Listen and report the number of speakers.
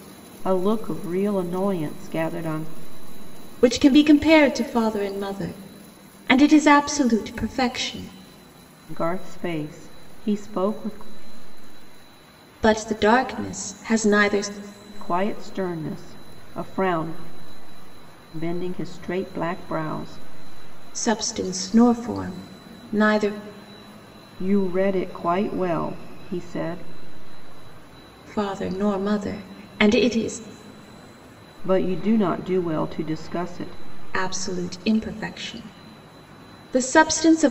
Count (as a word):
two